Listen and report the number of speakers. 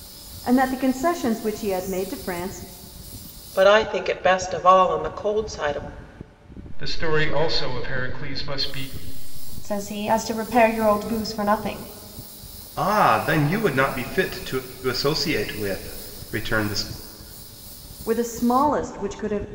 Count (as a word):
five